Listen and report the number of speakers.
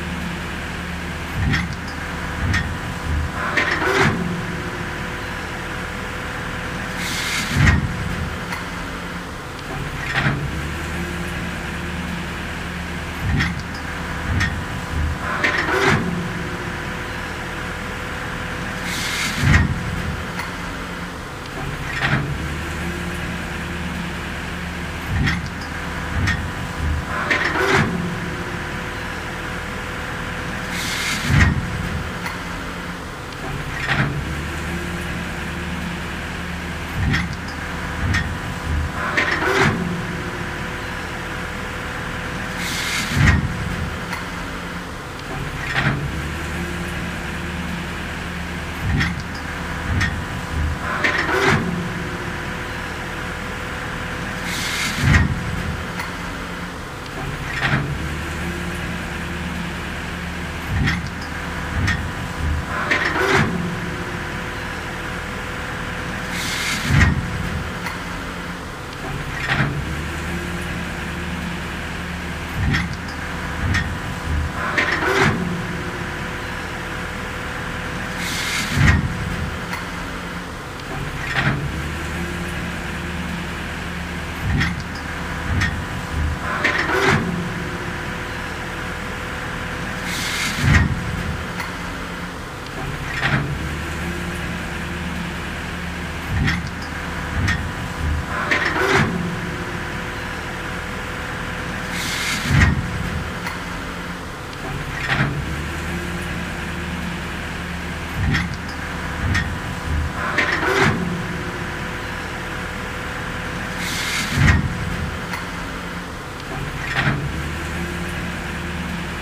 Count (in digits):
0